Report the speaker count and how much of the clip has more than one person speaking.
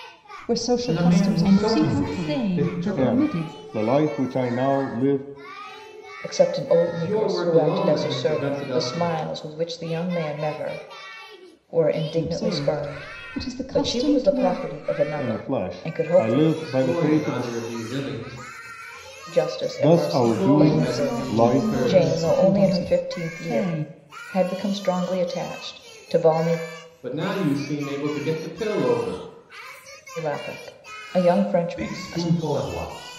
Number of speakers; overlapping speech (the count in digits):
6, about 42%